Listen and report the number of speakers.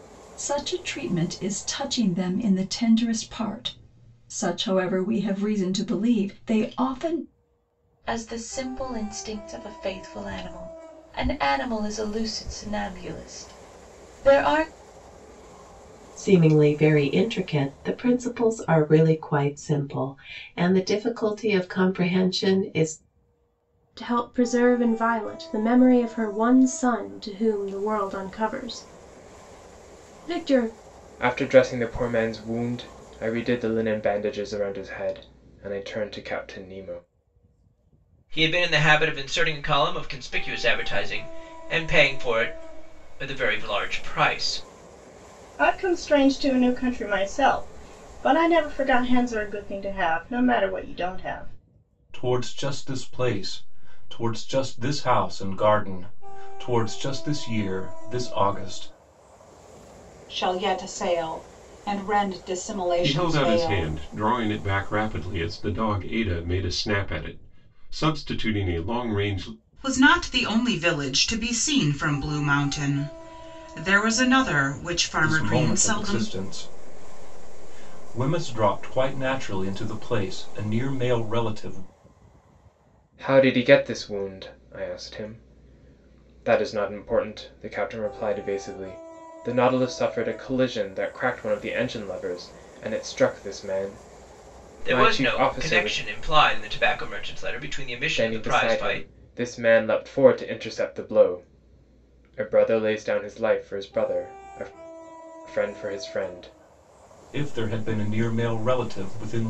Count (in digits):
10